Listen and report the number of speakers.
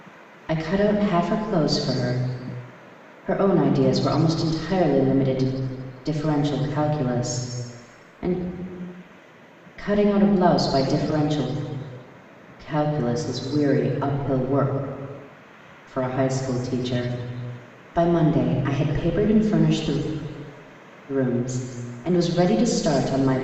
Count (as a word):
one